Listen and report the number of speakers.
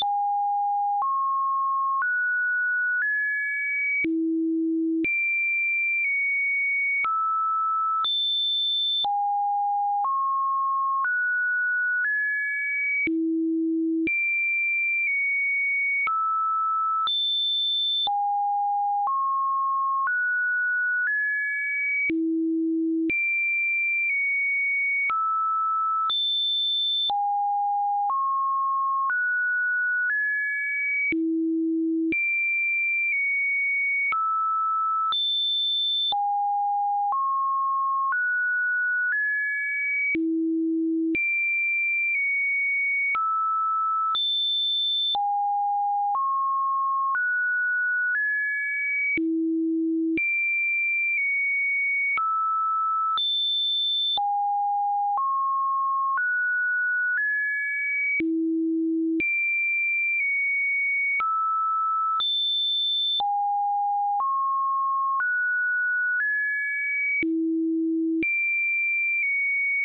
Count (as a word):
zero